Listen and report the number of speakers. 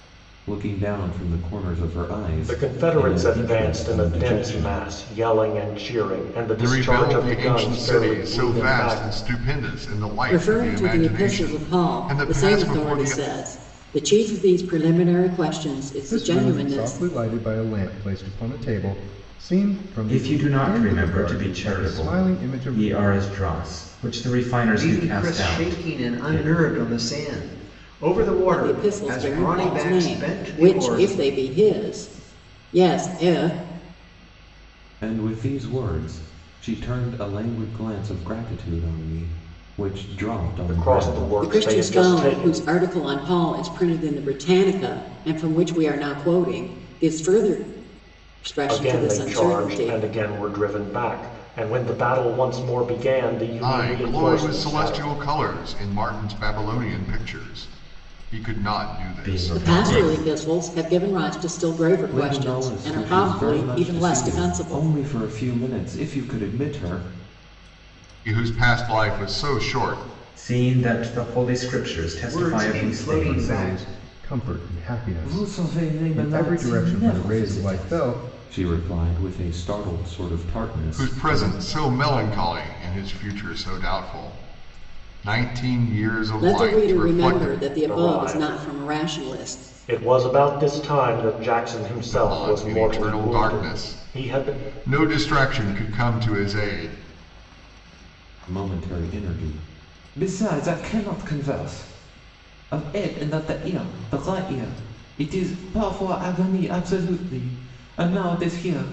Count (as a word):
seven